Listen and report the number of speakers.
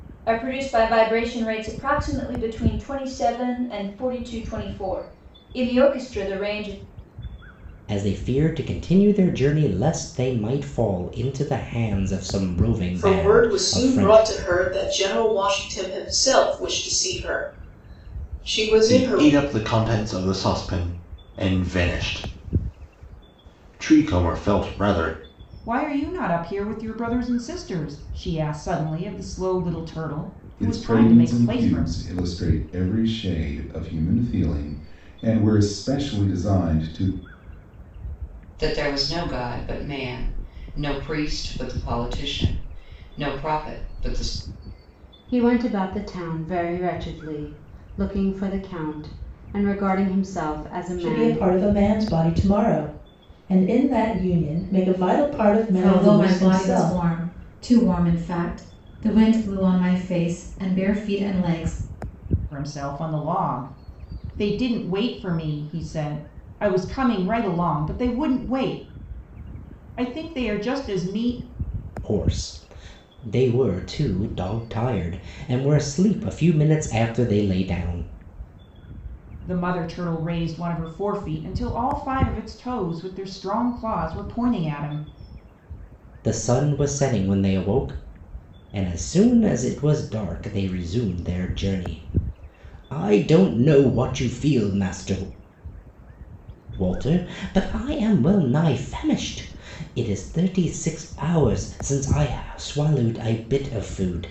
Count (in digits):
10